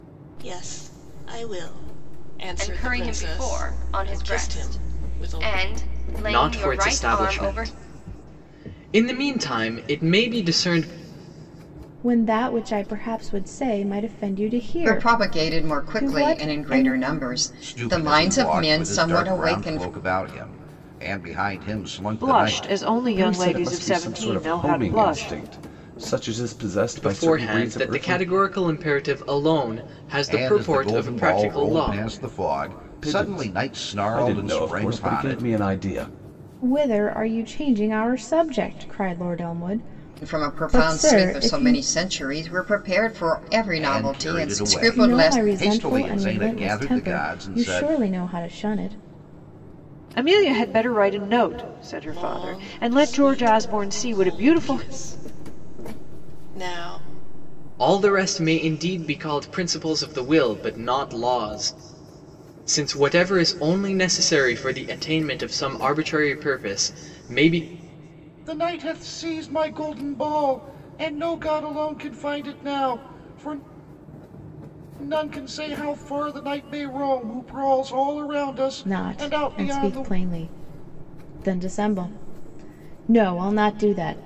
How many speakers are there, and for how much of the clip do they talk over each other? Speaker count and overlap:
8, about 32%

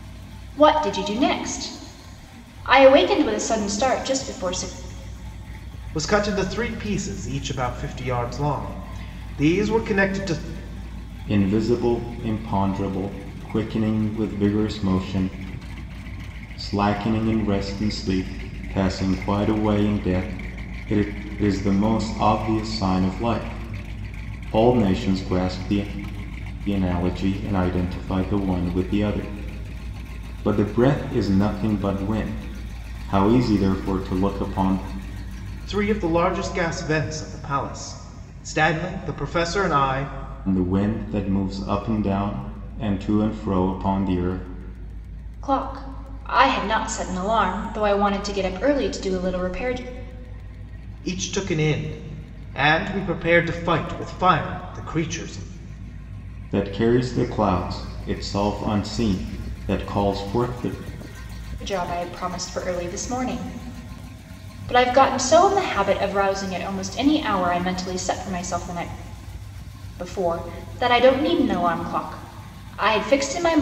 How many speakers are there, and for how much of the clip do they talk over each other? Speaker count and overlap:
3, no overlap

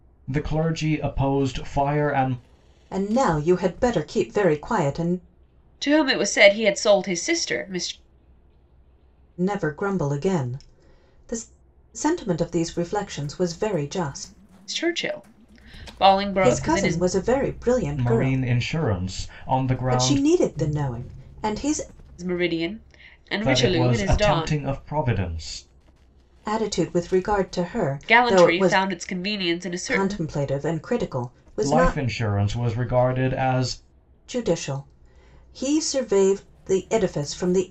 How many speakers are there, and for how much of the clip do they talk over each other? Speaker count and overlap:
3, about 12%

